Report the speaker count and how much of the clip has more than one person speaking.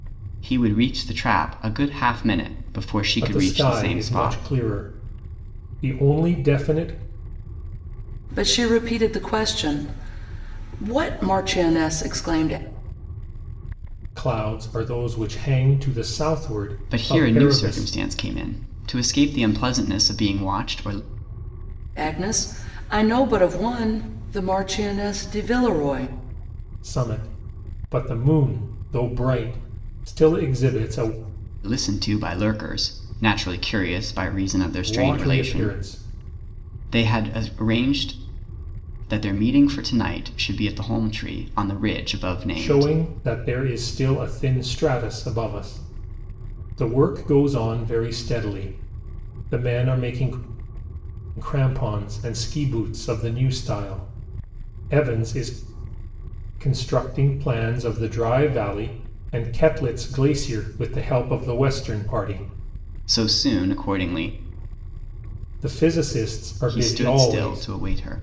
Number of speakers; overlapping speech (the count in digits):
3, about 7%